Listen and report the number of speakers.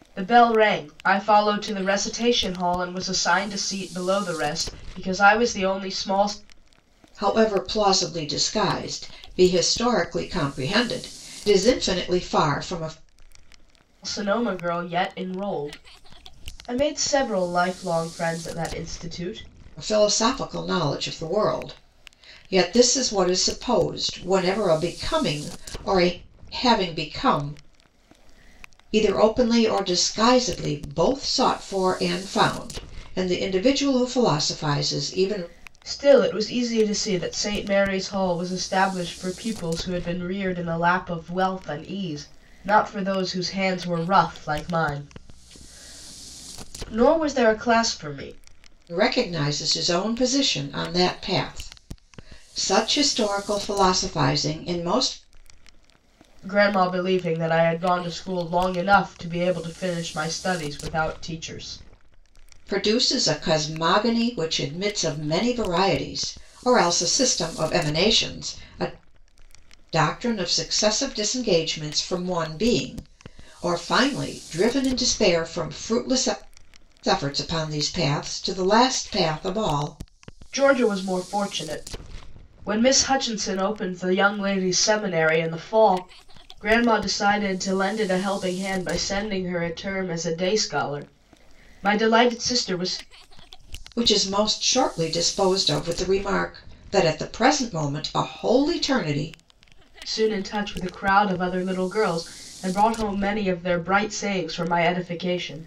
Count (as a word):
two